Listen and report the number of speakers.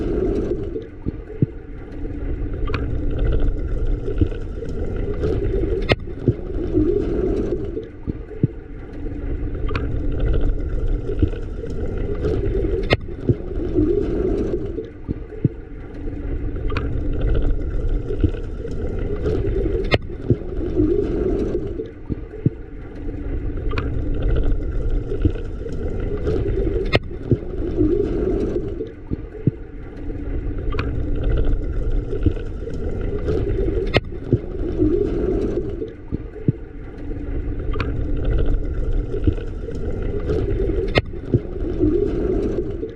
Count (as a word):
zero